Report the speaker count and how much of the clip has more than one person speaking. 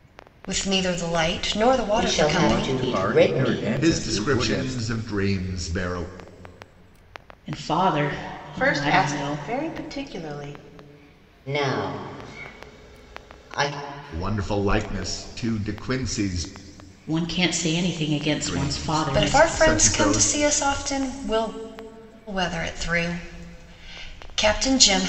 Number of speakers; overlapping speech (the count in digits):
6, about 23%